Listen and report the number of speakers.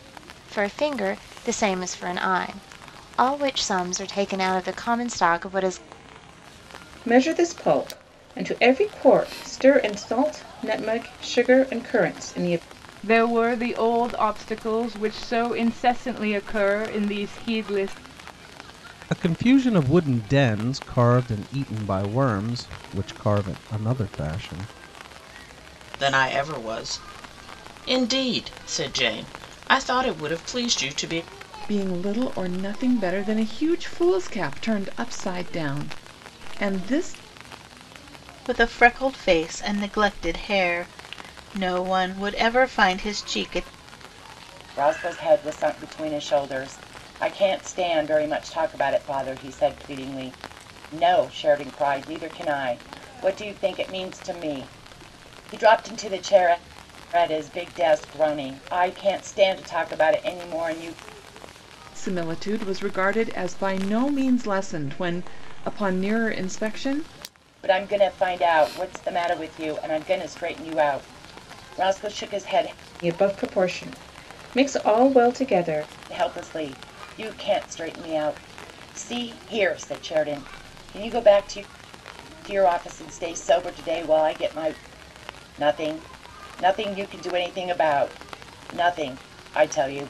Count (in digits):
8